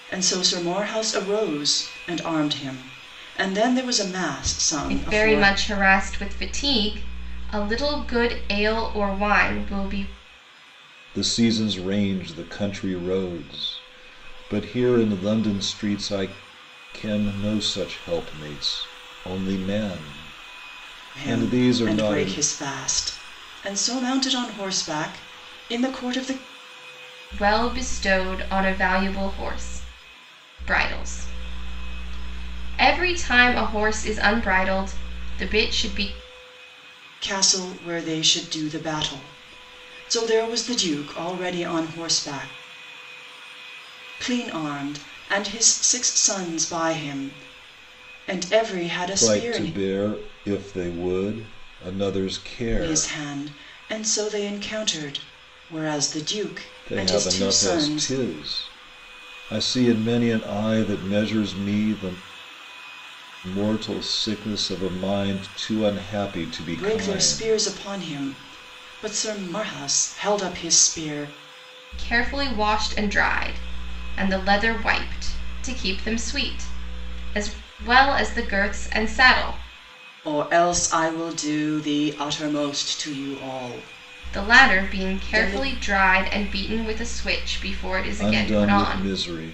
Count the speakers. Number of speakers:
three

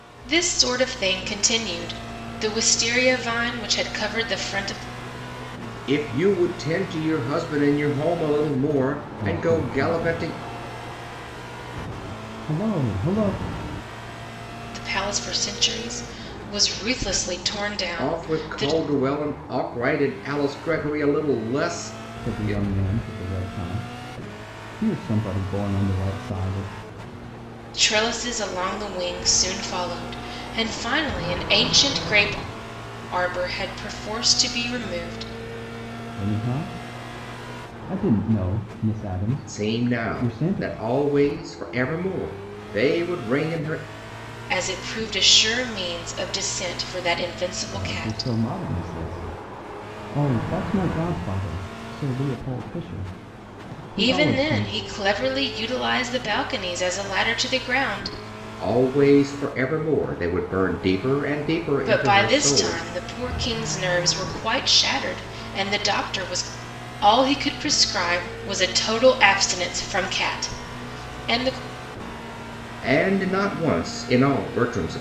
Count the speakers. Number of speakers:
three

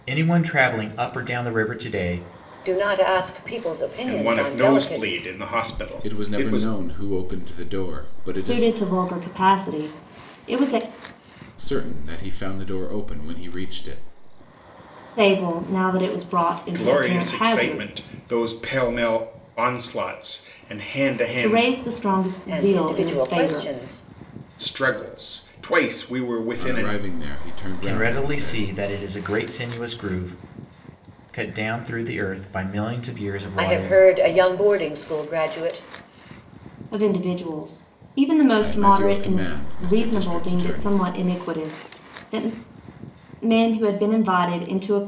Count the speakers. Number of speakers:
five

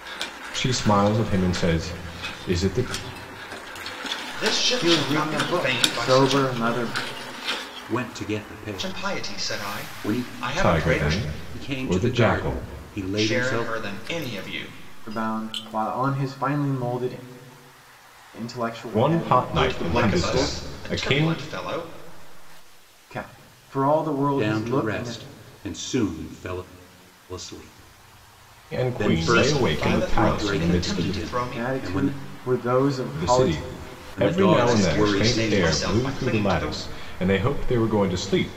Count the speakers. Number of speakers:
four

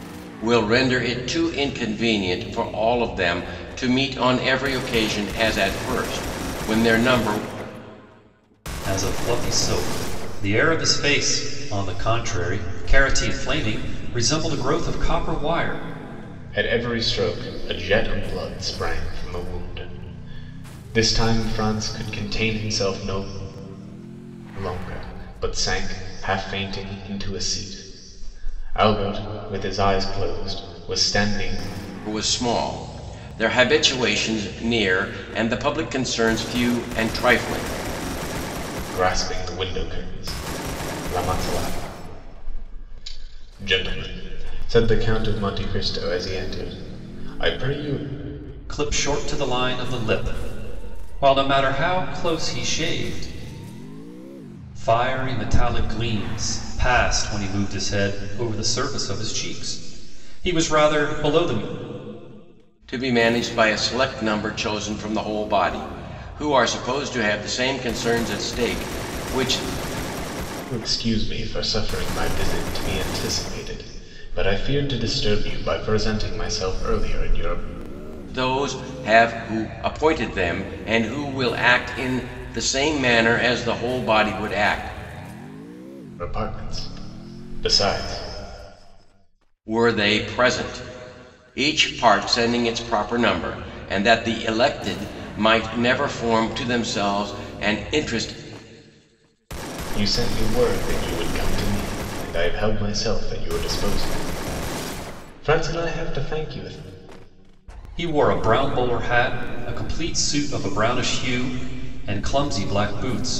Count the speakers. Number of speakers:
three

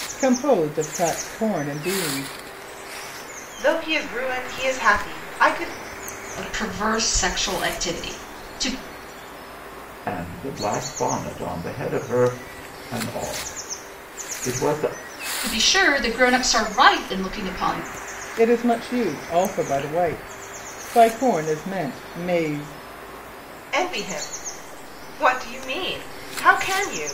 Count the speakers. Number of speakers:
four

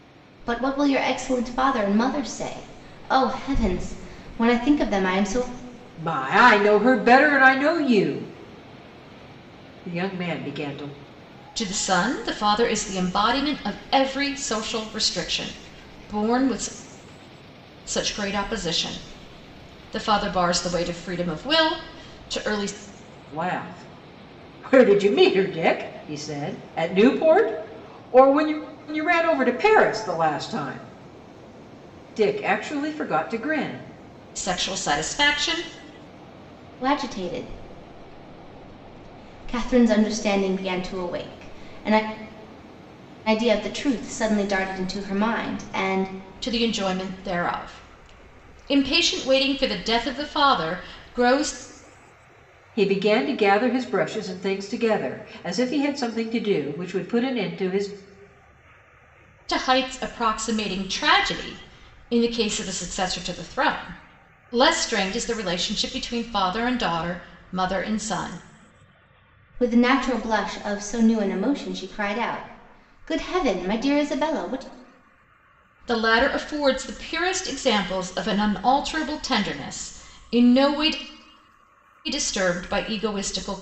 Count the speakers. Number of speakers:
three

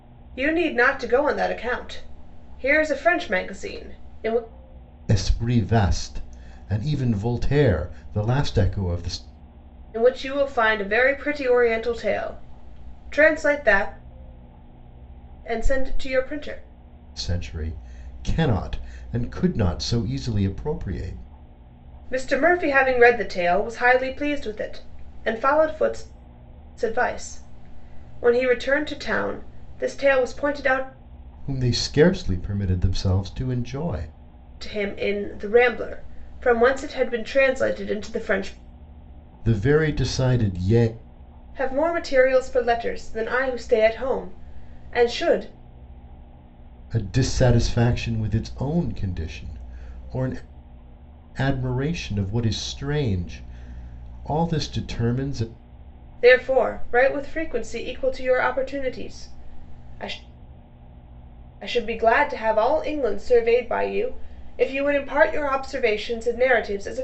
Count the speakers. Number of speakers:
two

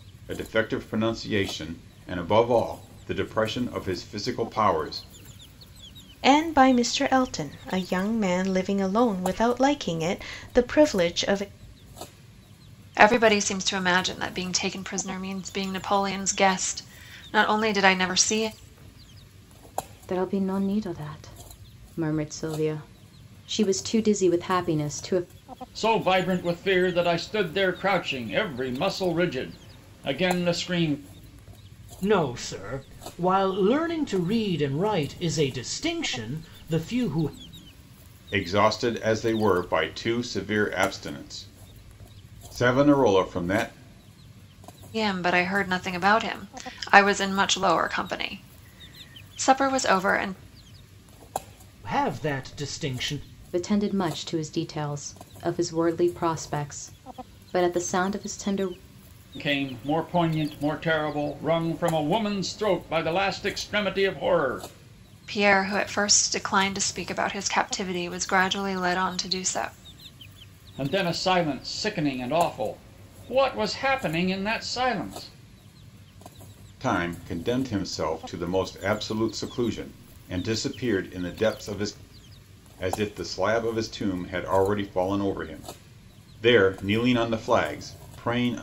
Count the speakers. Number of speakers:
six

